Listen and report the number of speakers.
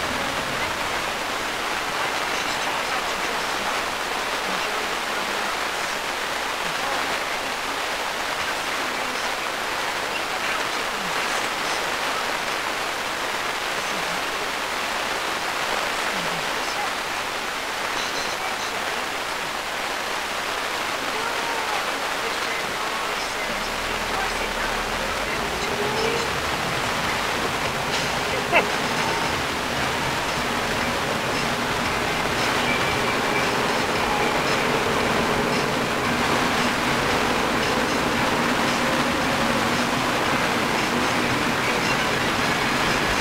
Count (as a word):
zero